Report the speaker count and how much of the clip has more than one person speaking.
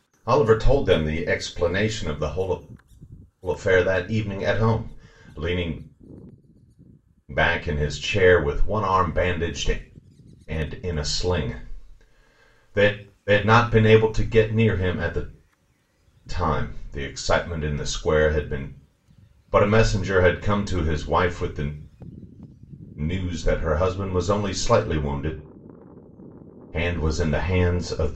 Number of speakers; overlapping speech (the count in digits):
1, no overlap